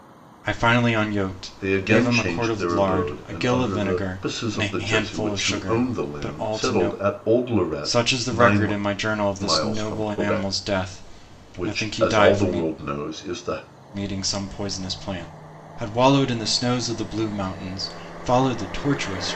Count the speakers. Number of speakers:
2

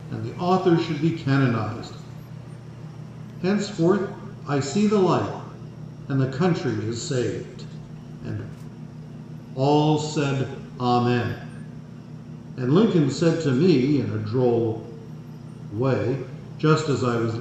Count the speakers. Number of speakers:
1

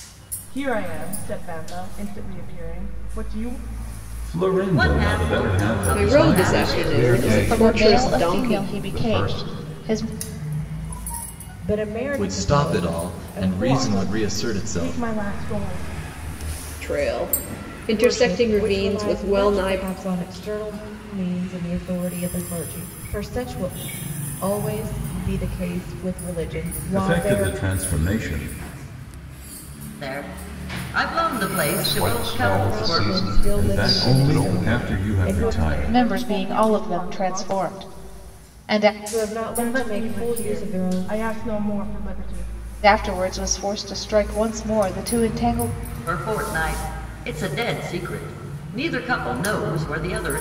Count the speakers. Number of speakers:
8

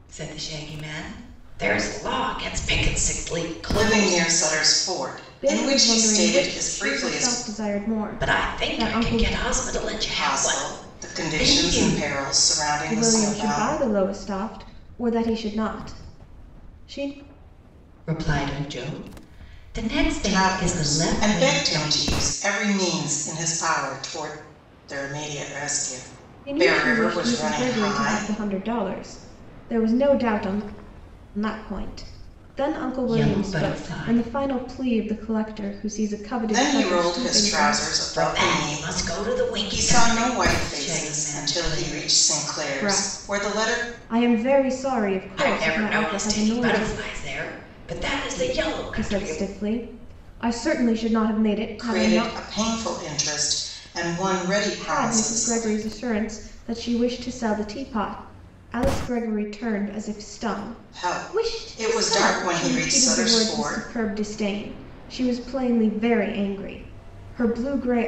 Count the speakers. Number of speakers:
3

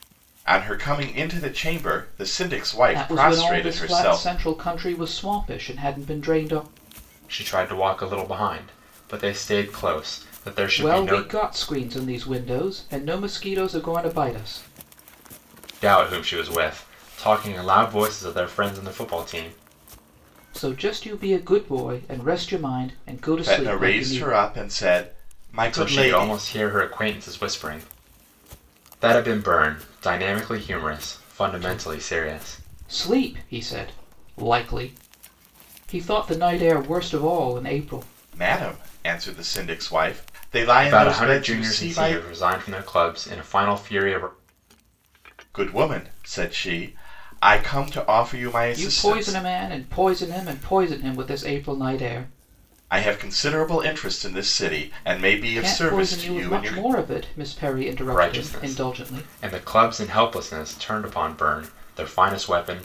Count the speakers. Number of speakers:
3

